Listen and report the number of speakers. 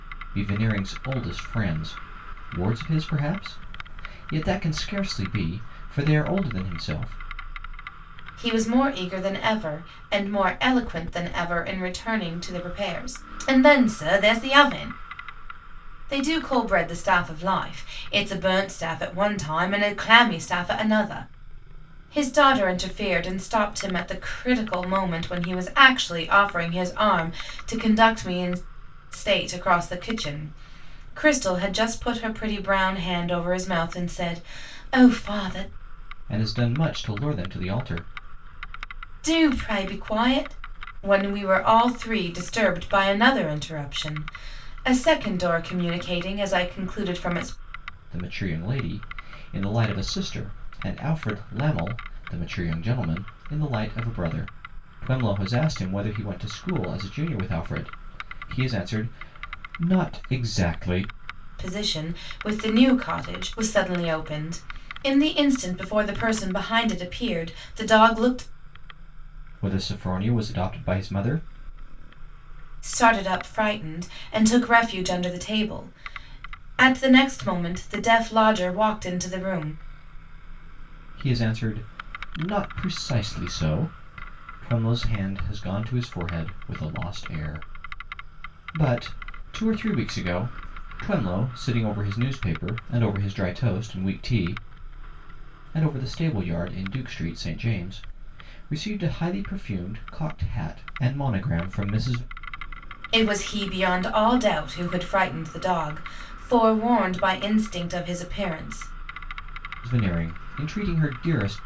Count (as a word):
two